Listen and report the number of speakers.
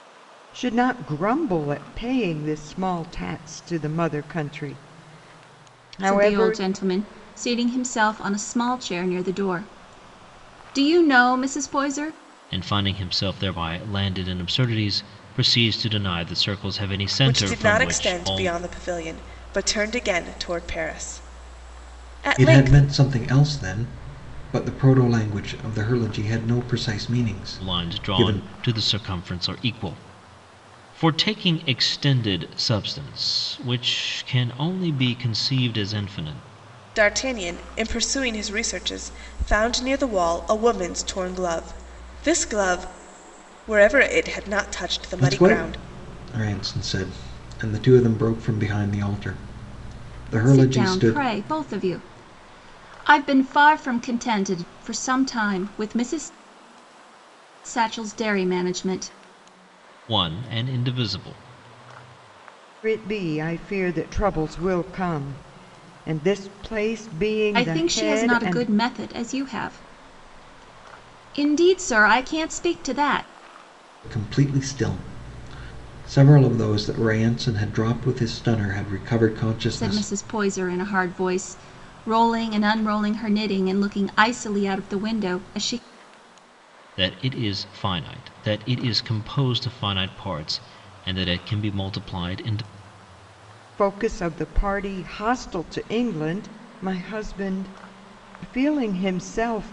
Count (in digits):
5